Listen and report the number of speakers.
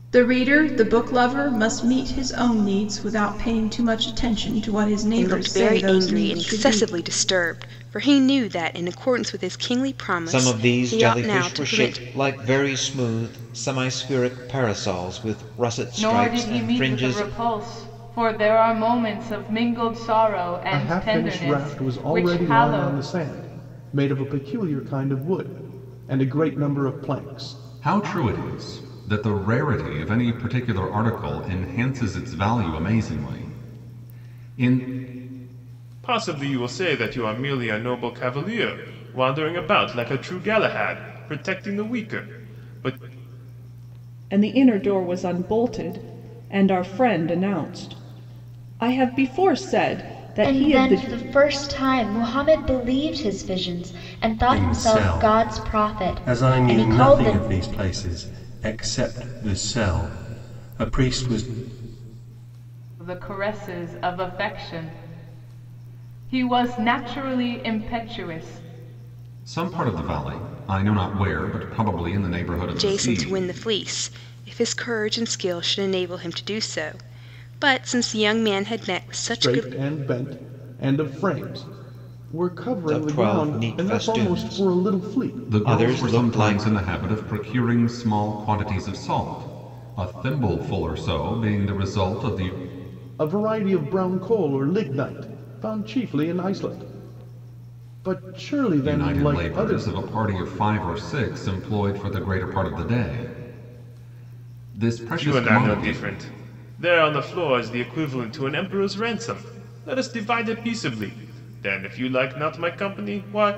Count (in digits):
10